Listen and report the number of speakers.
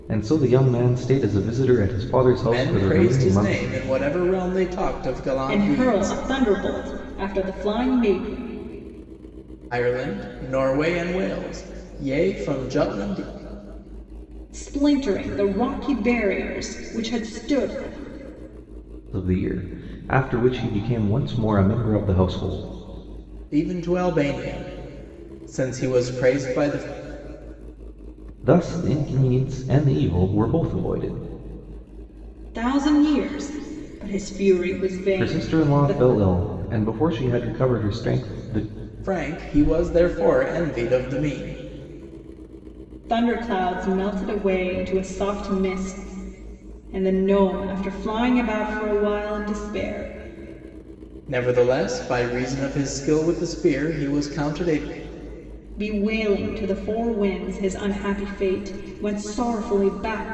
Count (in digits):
3